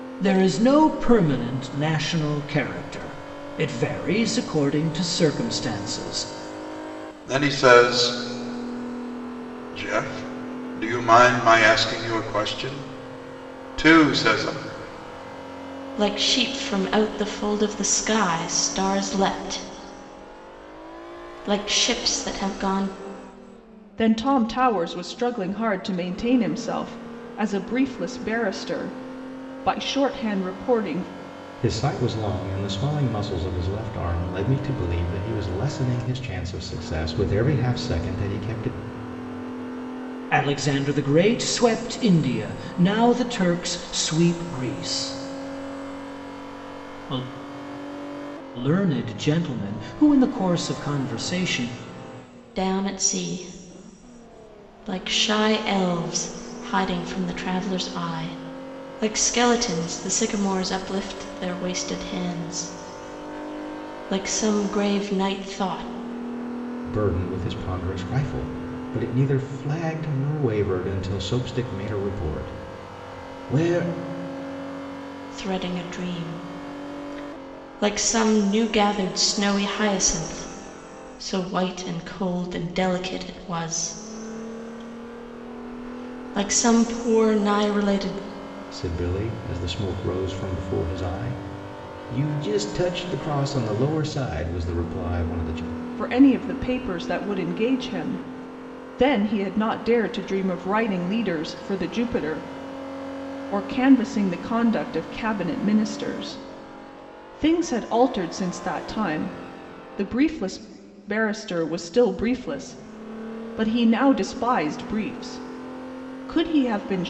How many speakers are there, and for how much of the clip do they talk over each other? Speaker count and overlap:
5, no overlap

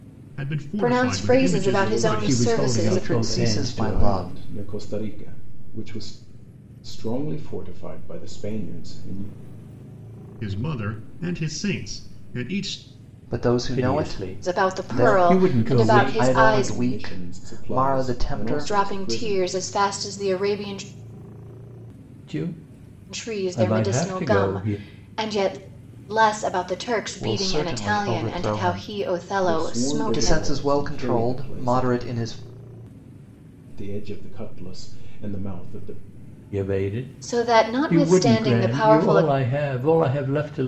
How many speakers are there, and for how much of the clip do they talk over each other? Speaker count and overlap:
5, about 43%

